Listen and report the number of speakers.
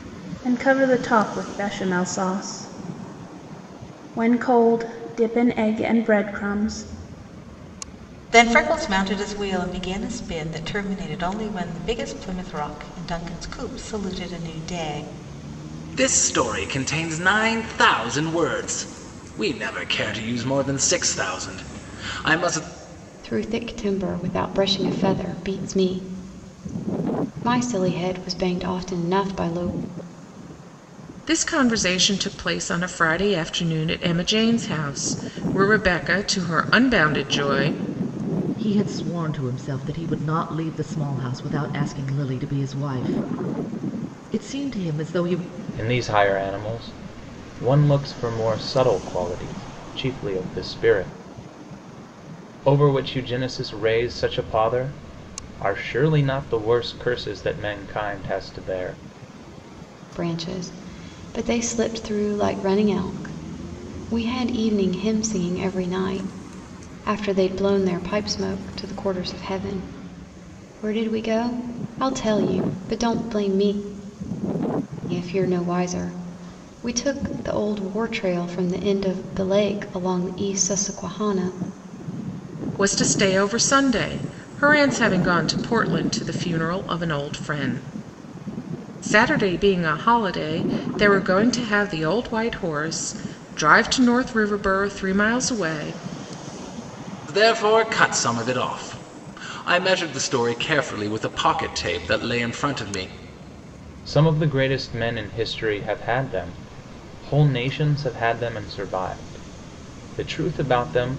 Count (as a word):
seven